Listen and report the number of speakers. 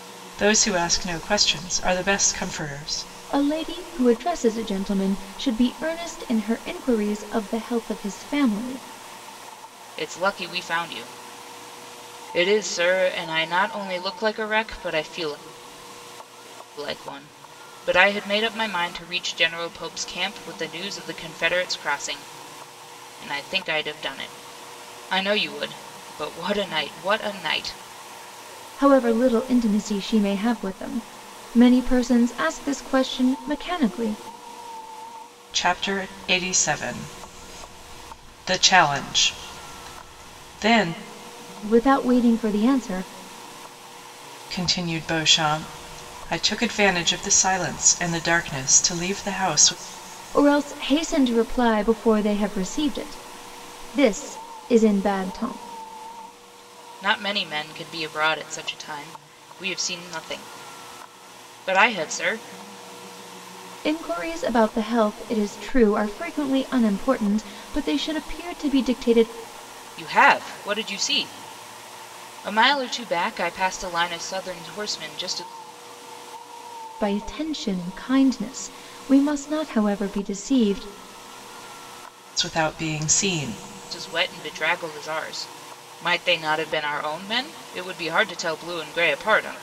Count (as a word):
three